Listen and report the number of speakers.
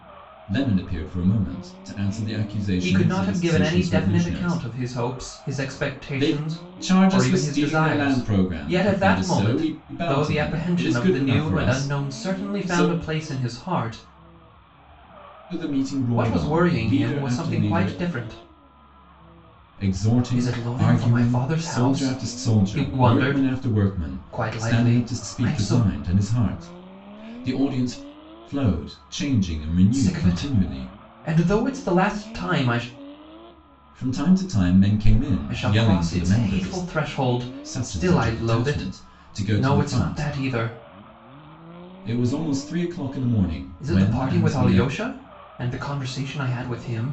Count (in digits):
2